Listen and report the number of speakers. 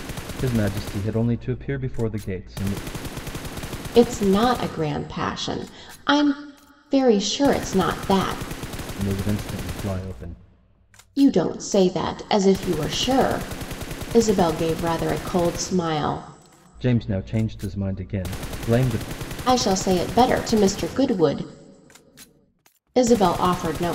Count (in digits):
2